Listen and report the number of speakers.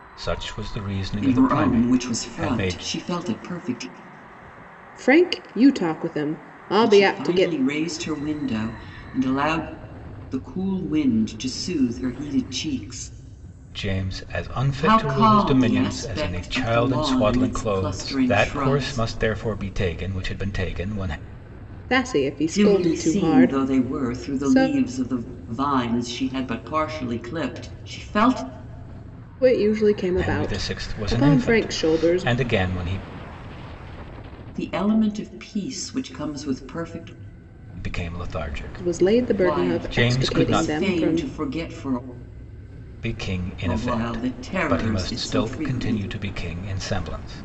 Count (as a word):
three